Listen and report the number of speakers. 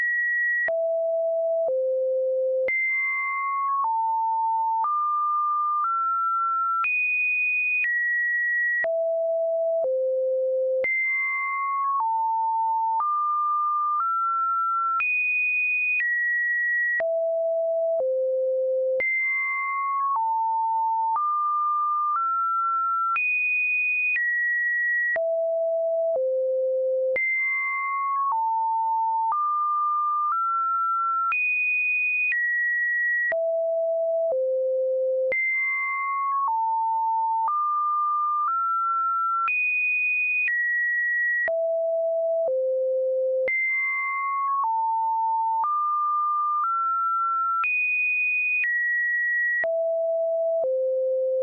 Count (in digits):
0